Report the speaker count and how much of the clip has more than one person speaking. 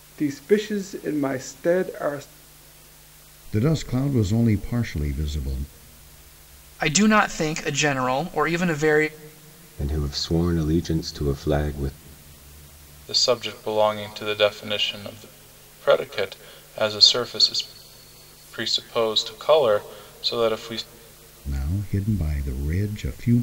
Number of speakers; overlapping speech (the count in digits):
5, no overlap